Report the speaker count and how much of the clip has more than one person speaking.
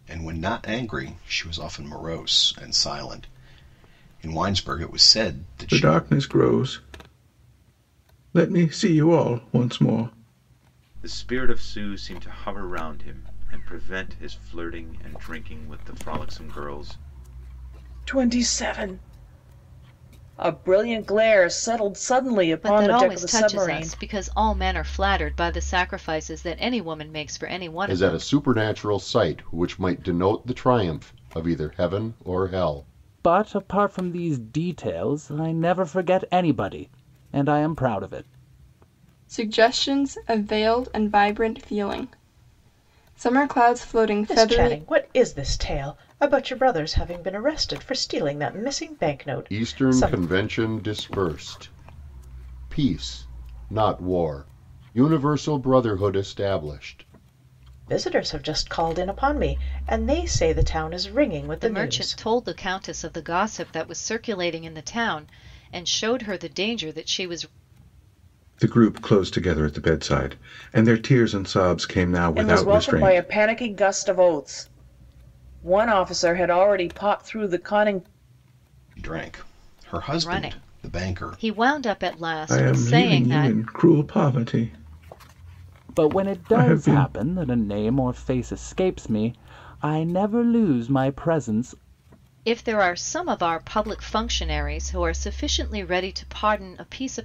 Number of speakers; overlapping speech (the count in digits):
9, about 9%